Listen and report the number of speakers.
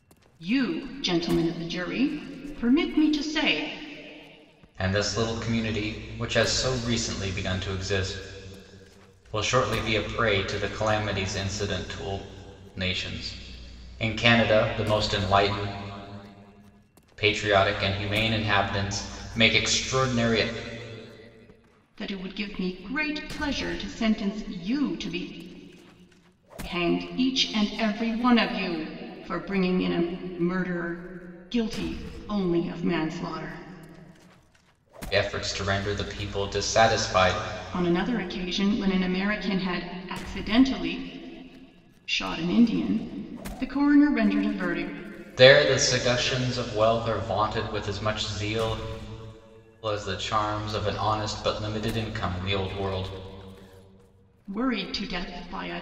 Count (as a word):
two